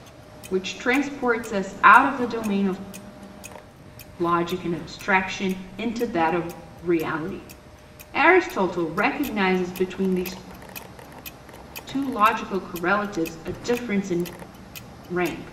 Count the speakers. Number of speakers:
1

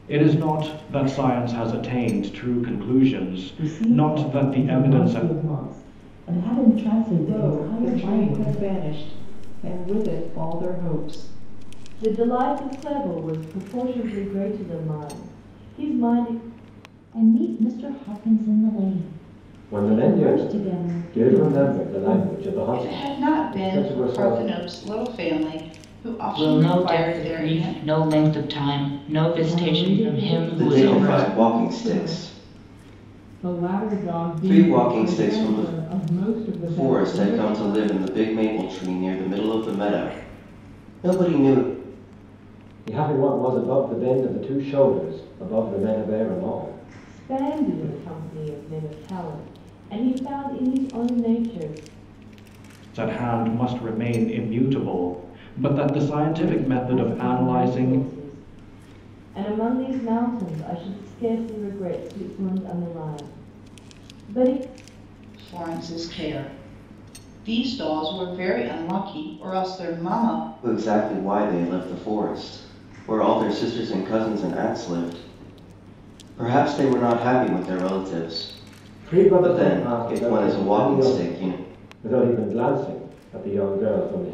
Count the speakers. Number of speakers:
10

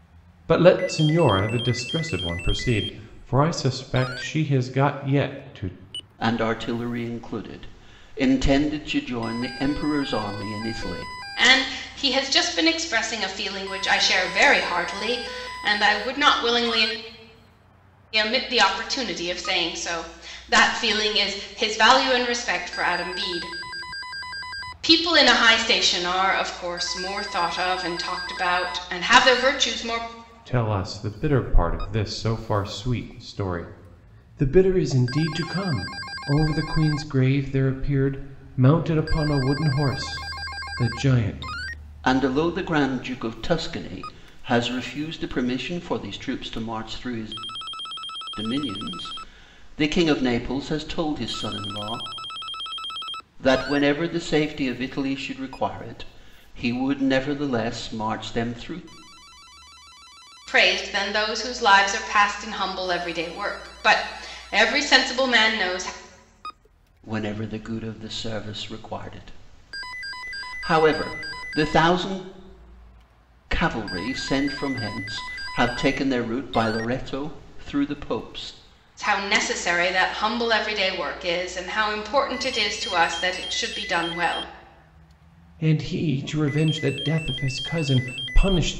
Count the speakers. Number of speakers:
3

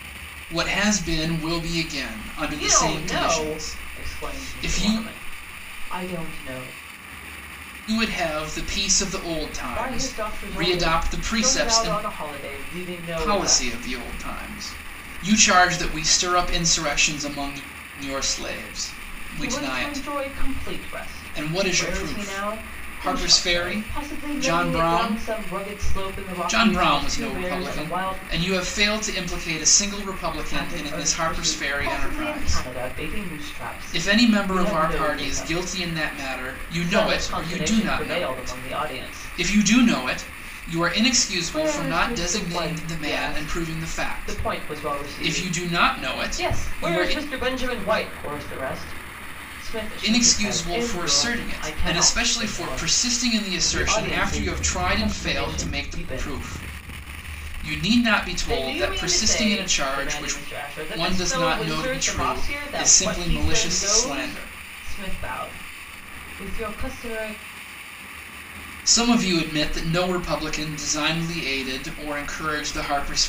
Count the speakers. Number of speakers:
2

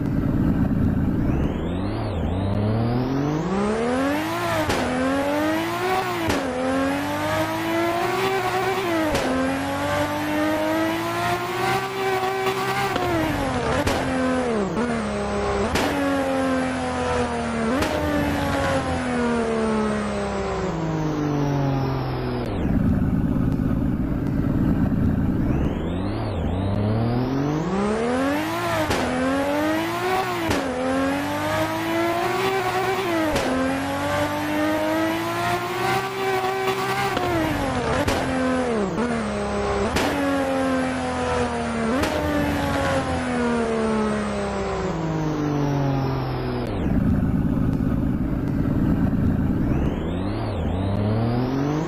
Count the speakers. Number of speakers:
0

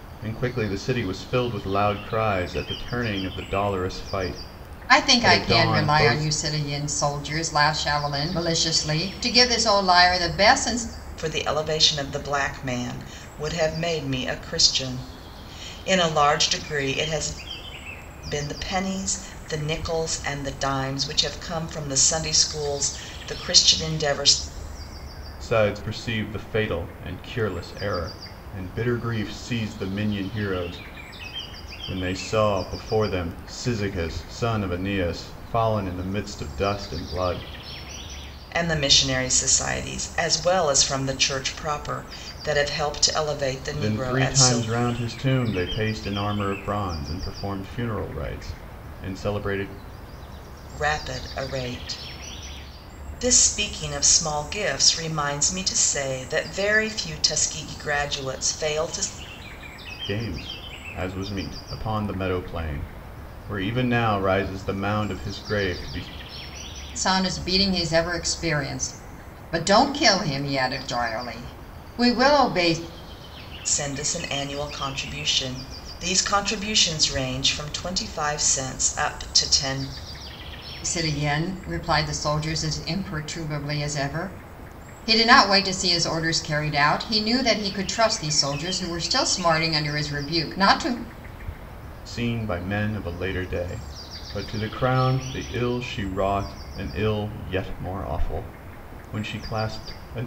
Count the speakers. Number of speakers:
3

